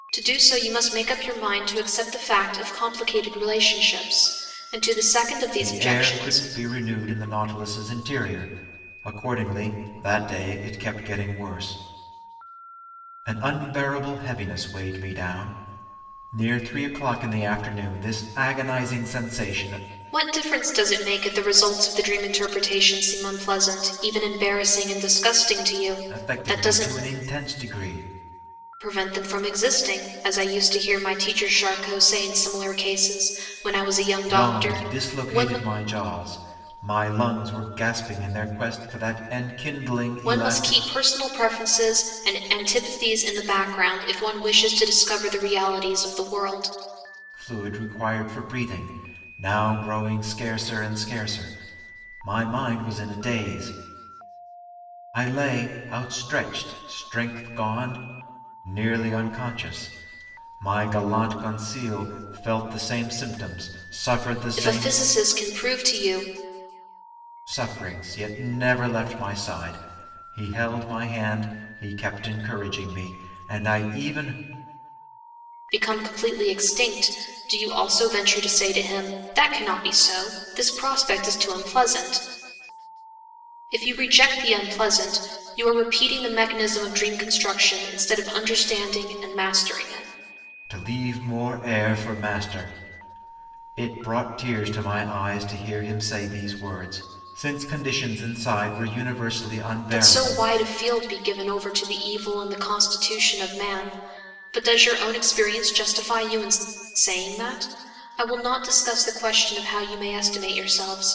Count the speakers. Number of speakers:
2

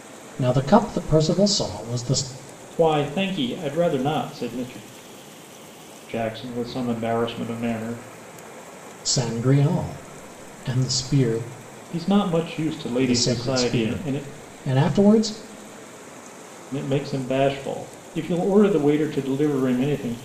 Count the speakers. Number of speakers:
2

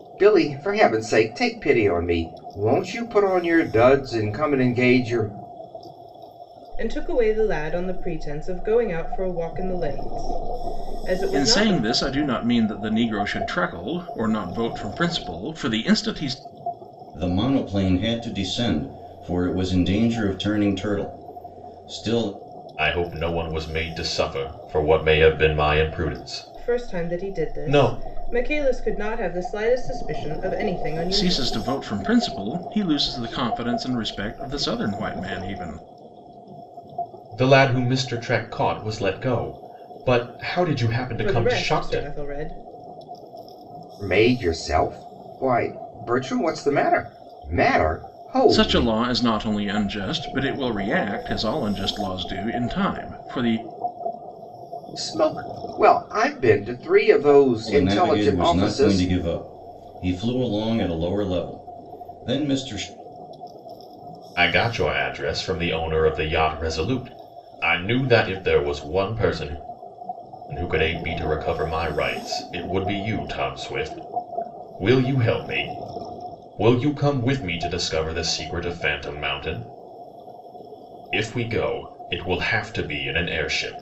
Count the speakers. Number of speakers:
5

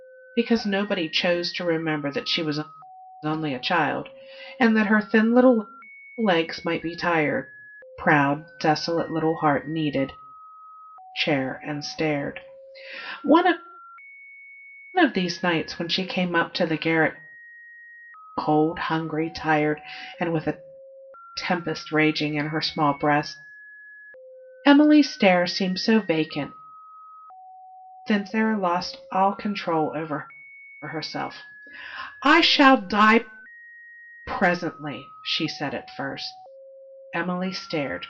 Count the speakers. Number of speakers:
1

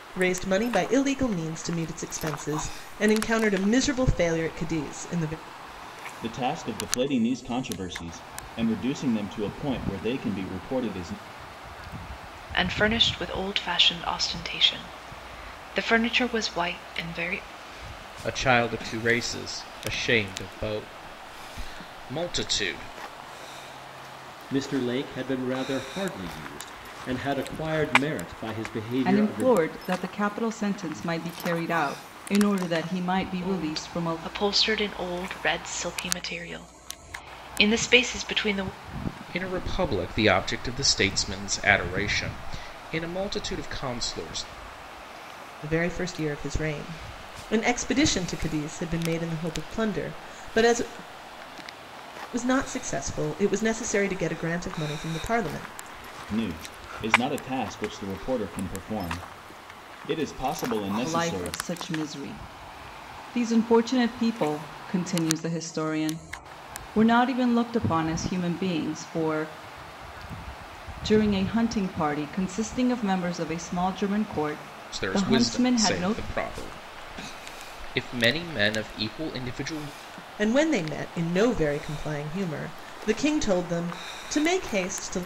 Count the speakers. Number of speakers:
6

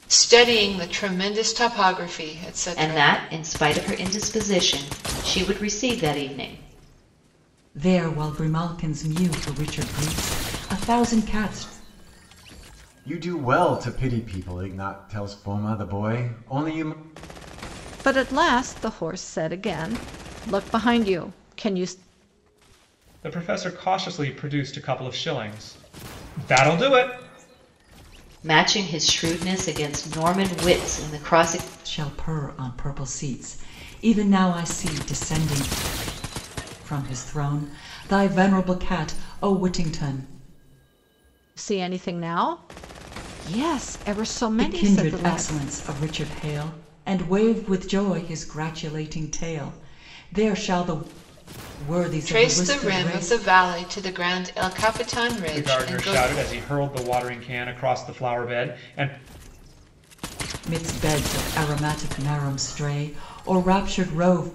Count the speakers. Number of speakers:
6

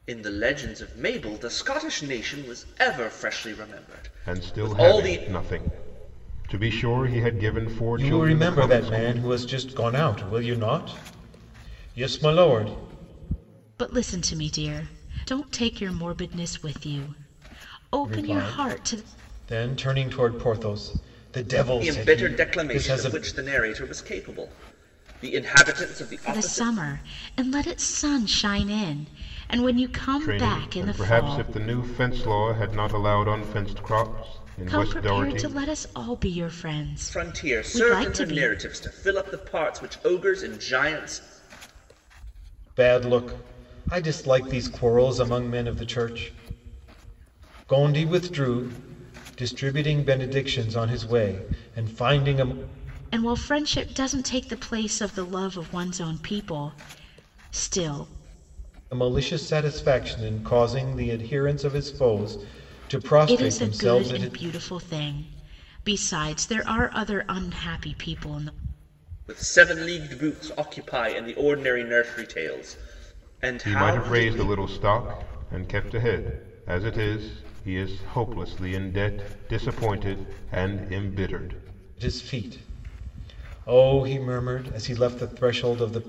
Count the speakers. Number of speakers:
4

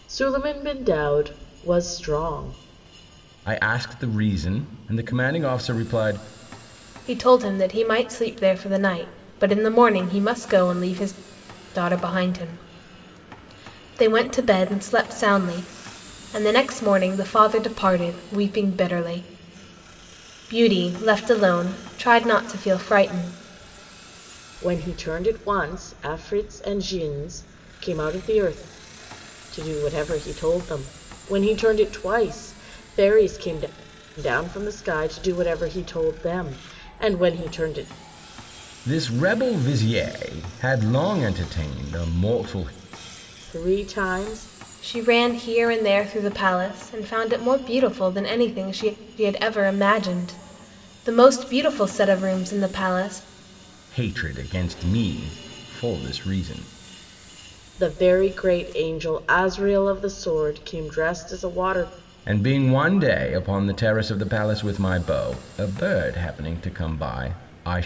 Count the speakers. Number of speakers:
3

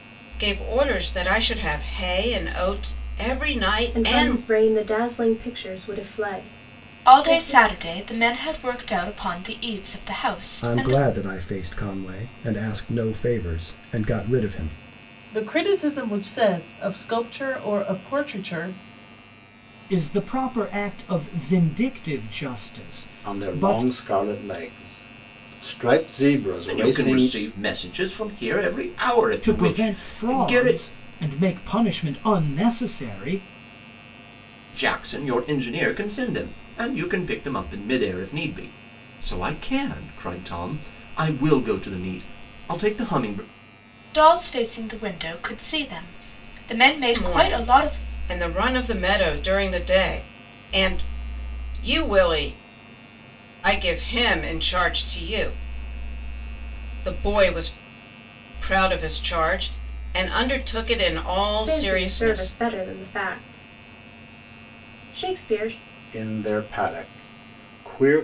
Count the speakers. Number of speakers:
8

